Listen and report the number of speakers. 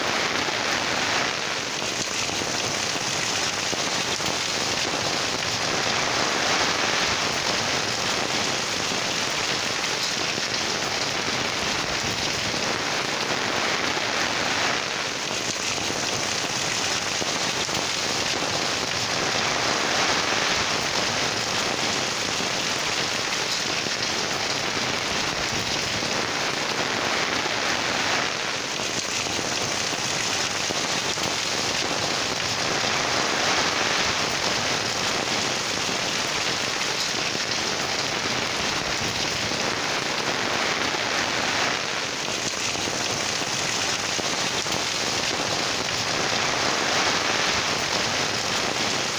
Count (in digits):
0